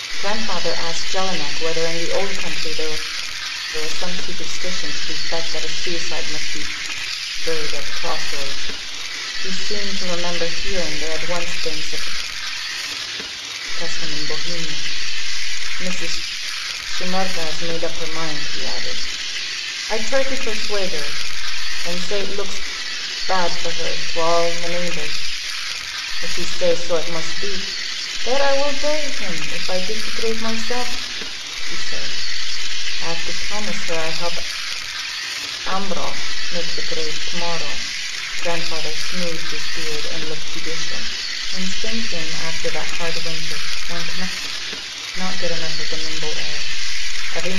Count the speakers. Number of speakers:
1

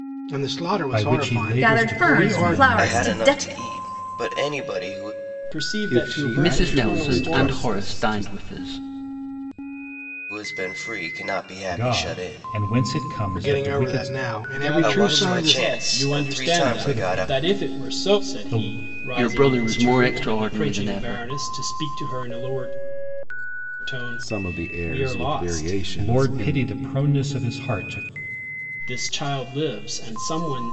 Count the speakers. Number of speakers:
7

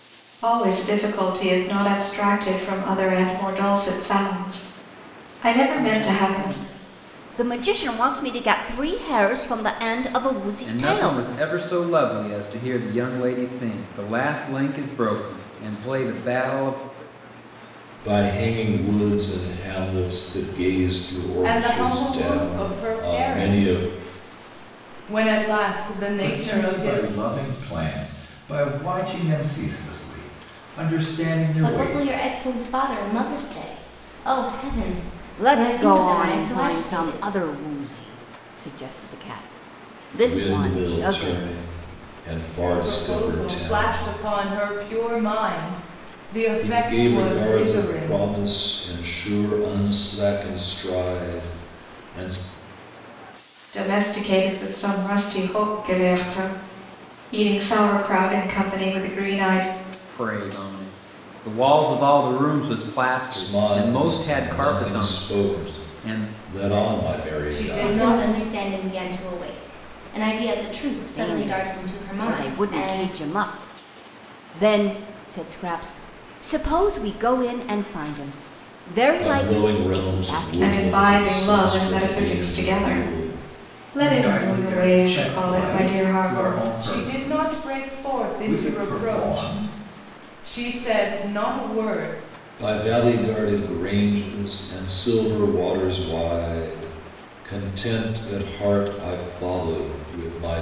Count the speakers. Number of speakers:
7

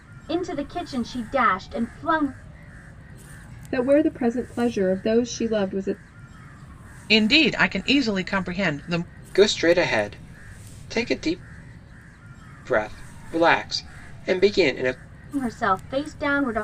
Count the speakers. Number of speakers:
4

